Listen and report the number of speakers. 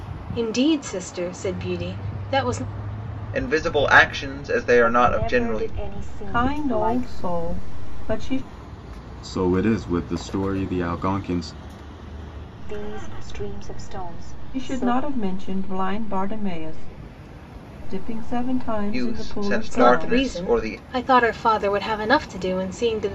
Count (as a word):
five